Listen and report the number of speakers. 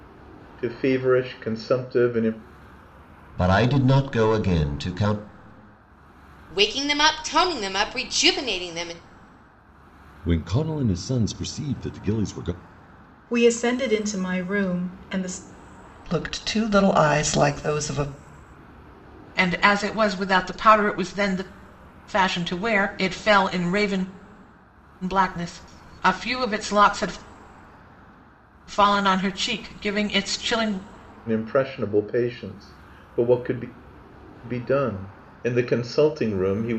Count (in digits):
7